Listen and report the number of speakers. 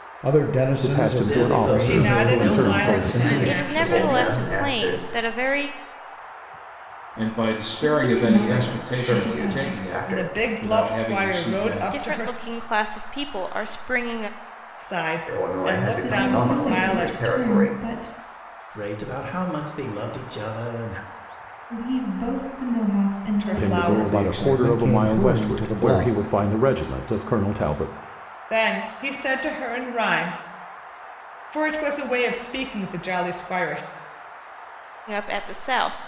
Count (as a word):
nine